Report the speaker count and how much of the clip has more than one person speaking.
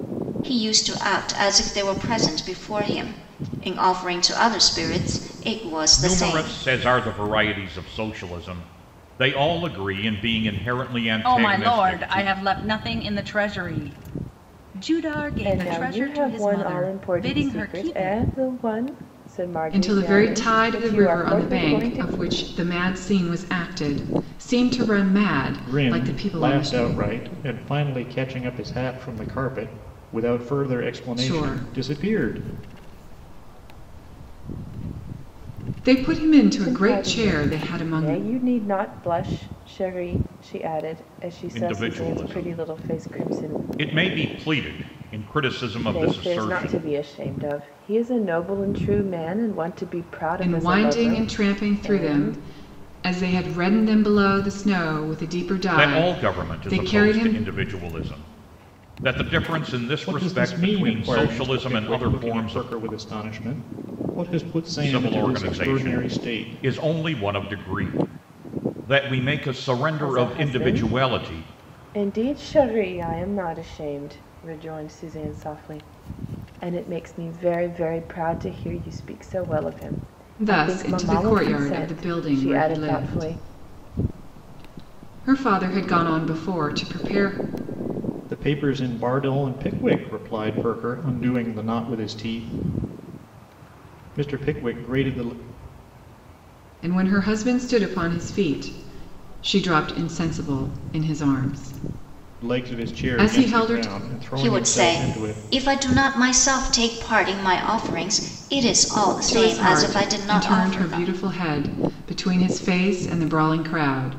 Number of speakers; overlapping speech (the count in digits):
6, about 28%